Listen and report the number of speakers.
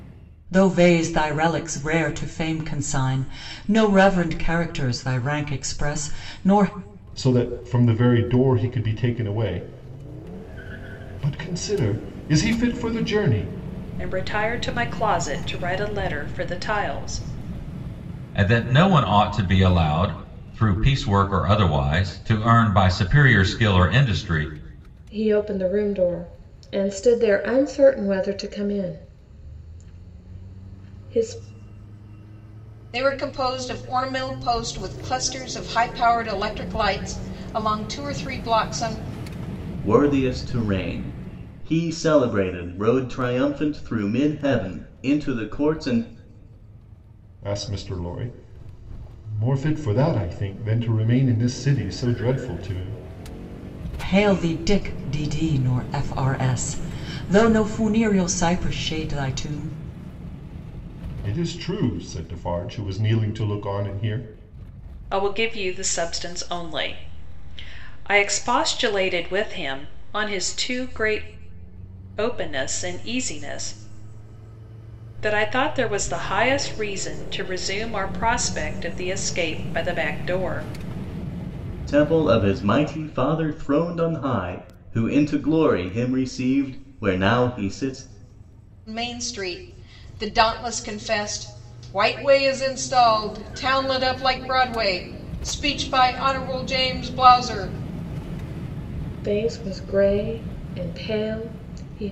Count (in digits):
7